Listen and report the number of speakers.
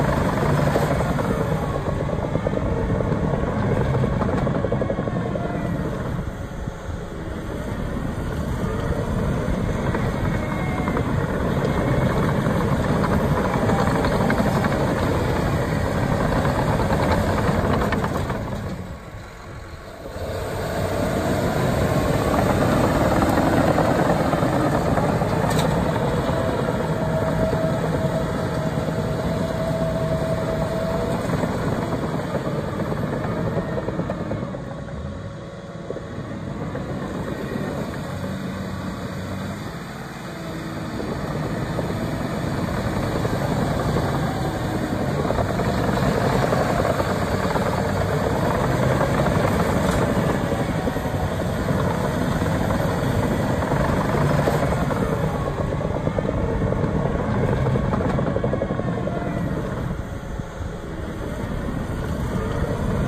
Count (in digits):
0